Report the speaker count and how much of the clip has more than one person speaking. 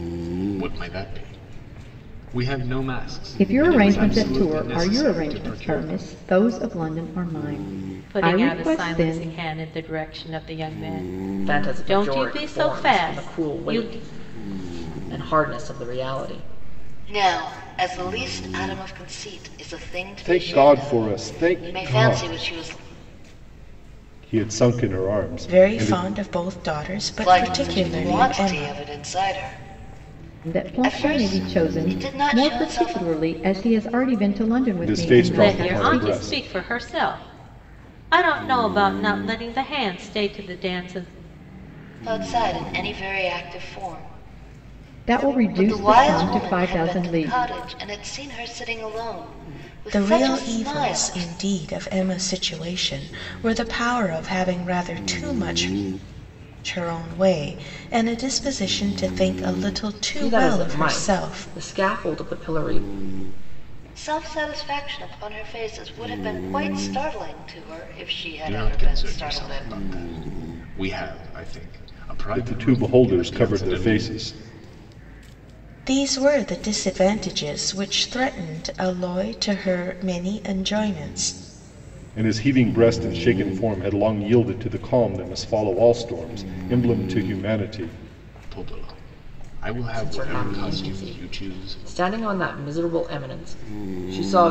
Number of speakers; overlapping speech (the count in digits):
7, about 27%